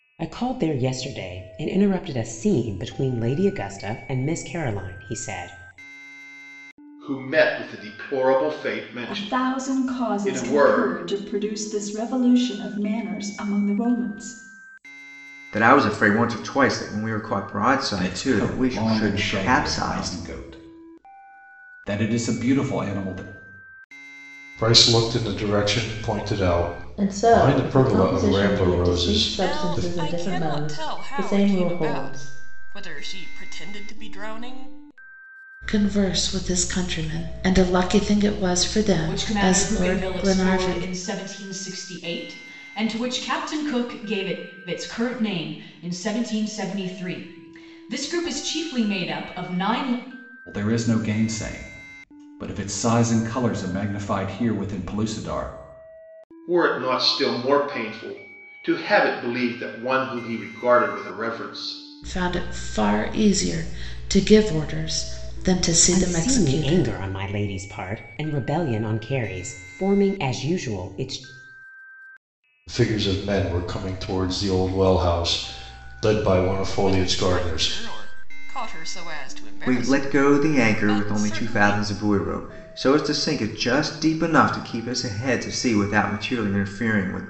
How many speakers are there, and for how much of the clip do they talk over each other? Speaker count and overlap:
ten, about 19%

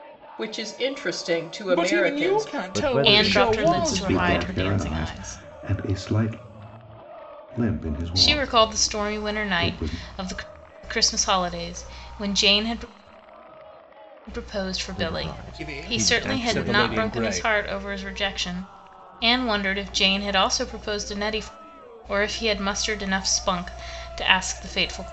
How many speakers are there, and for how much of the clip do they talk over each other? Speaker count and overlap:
five, about 32%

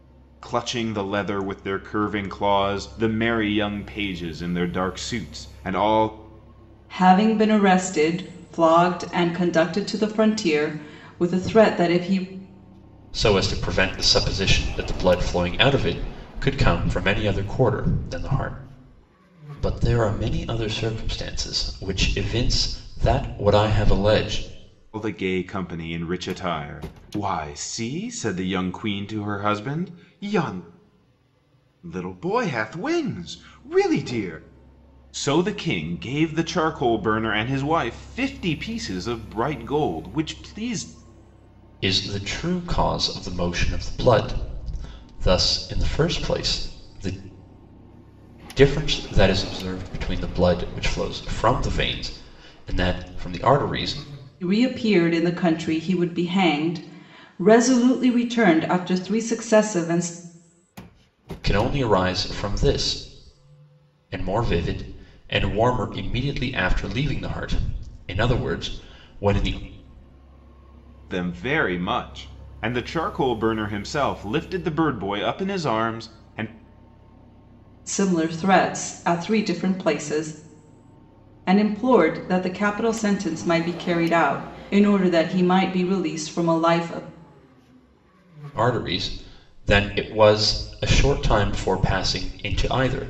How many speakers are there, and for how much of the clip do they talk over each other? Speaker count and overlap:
three, no overlap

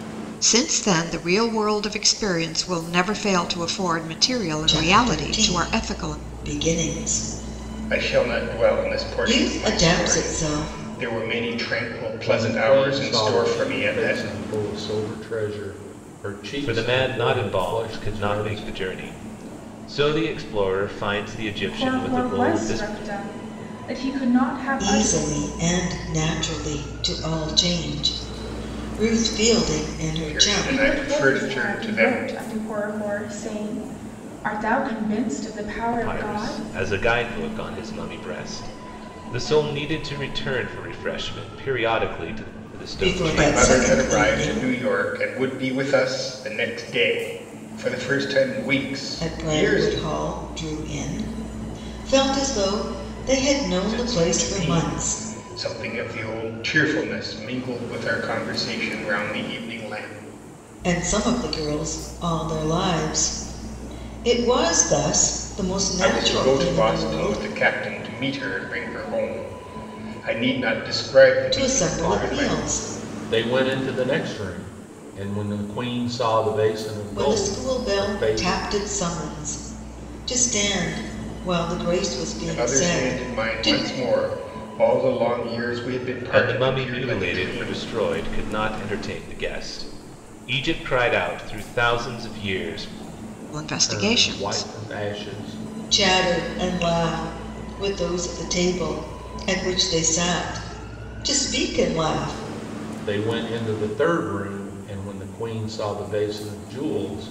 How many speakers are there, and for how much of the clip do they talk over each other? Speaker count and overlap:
six, about 24%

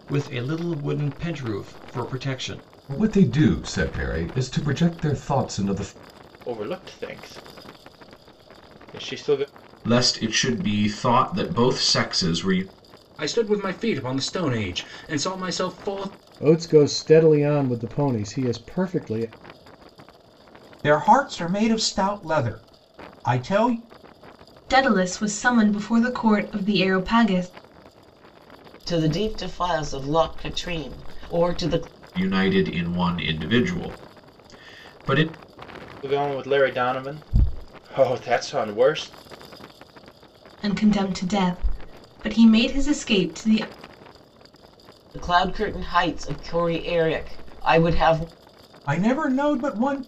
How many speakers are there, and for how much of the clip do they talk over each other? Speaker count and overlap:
nine, no overlap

